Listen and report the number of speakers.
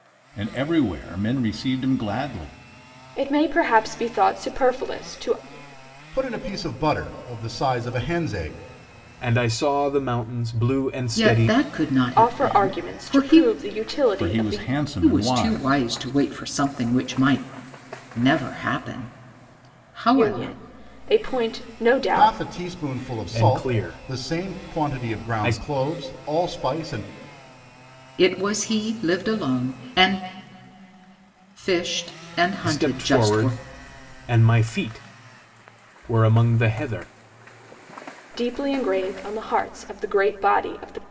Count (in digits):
5